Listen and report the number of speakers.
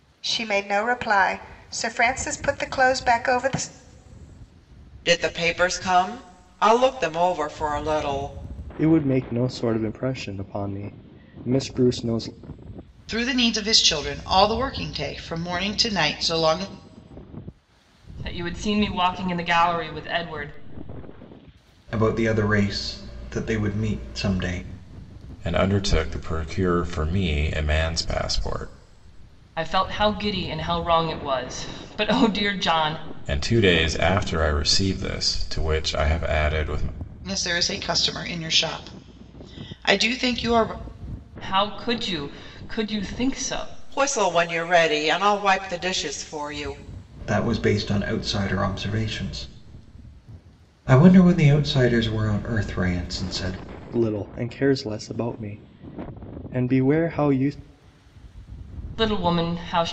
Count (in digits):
7